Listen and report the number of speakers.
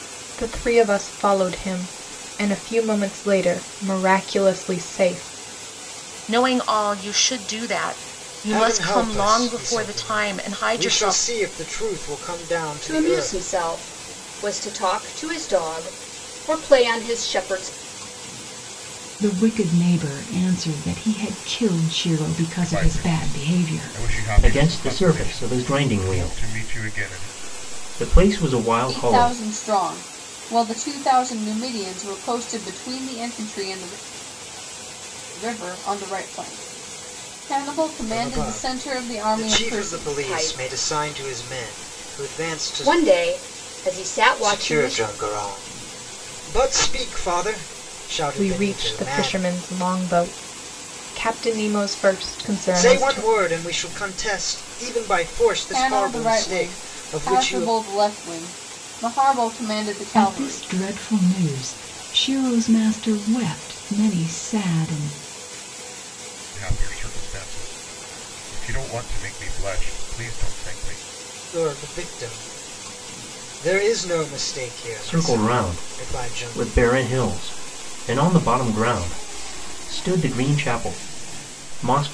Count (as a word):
eight